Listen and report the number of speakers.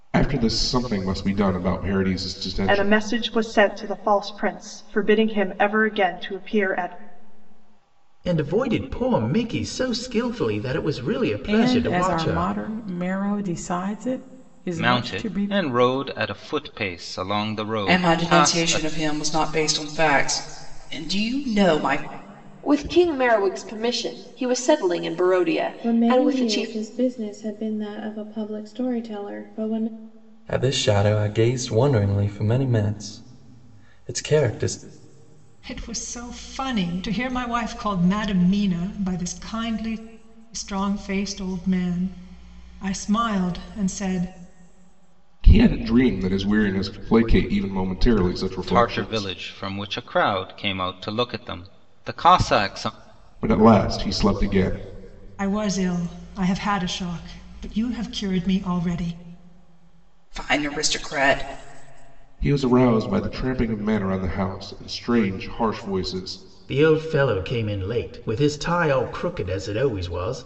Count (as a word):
ten